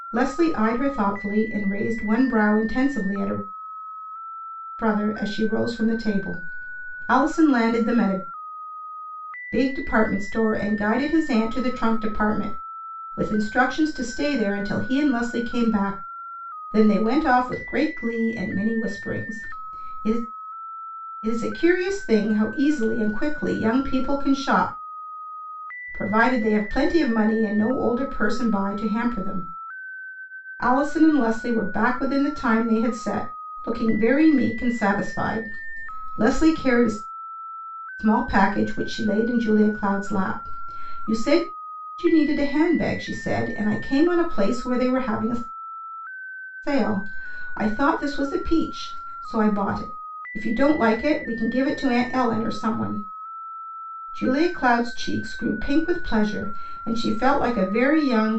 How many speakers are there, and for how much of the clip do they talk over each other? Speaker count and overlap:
1, no overlap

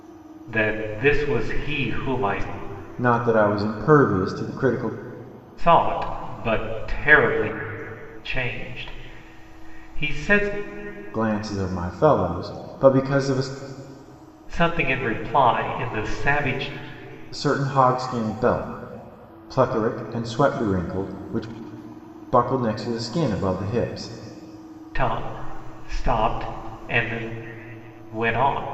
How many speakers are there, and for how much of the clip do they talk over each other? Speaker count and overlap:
2, no overlap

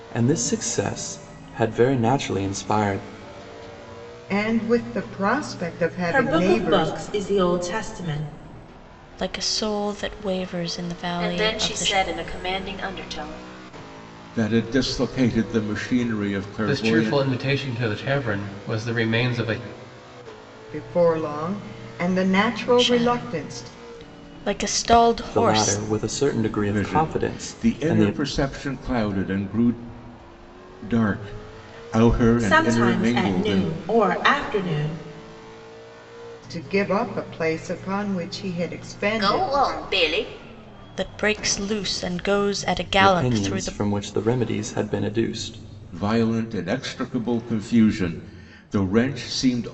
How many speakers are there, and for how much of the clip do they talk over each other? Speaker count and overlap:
7, about 16%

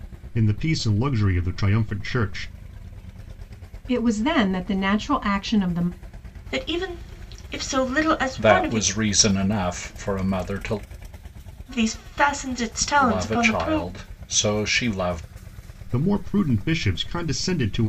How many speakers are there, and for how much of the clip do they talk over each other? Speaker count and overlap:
4, about 8%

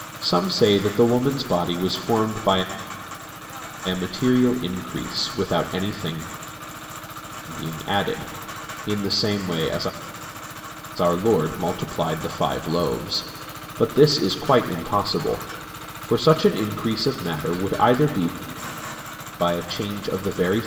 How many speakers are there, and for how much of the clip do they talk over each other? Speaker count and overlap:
1, no overlap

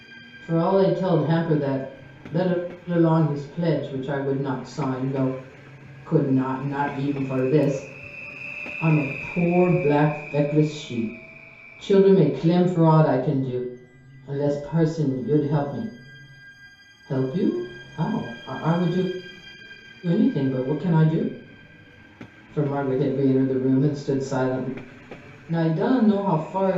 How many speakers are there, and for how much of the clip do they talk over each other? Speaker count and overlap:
1, no overlap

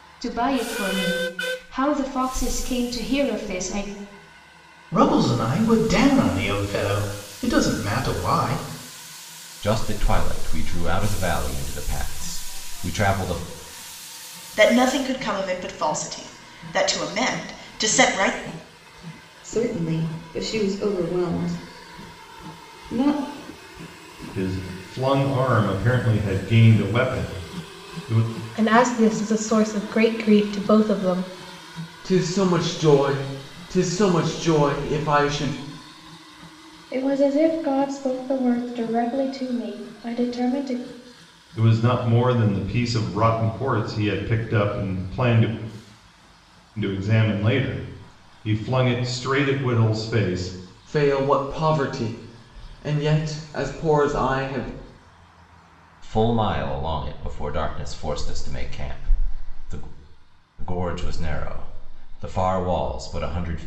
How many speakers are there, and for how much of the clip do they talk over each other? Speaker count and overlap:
9, no overlap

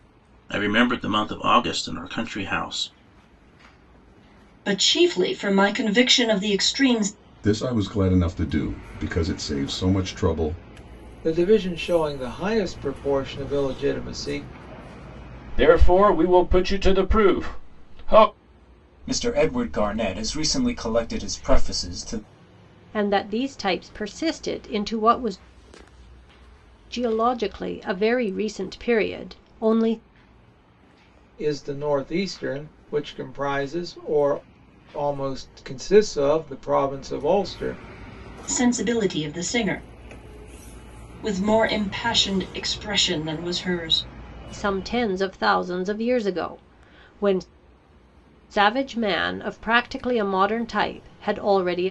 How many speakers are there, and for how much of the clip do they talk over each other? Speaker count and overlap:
7, no overlap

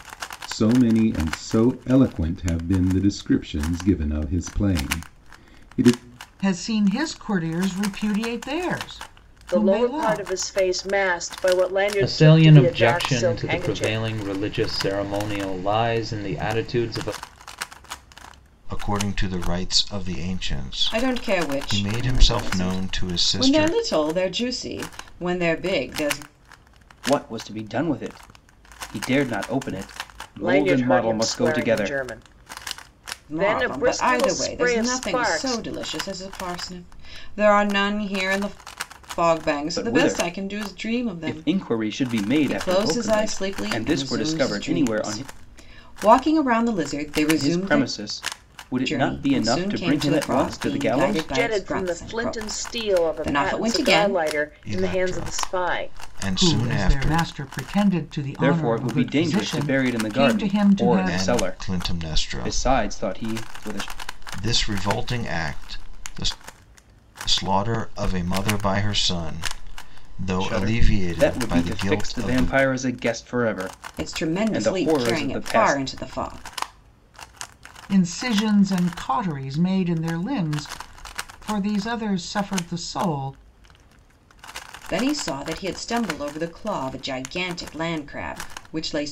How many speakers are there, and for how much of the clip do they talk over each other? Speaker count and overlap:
7, about 36%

